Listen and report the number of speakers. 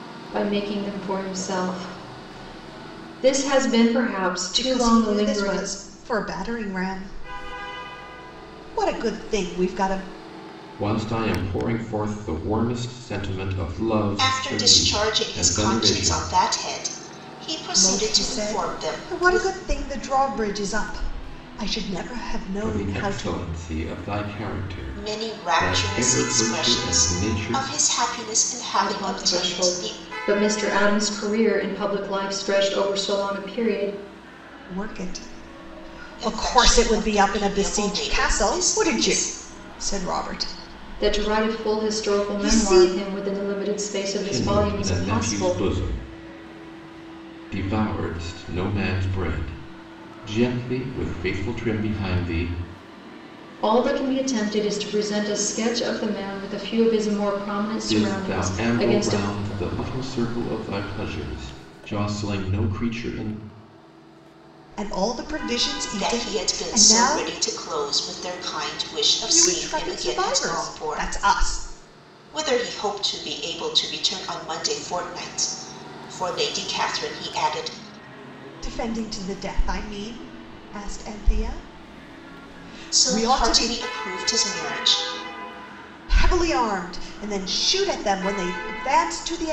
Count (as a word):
four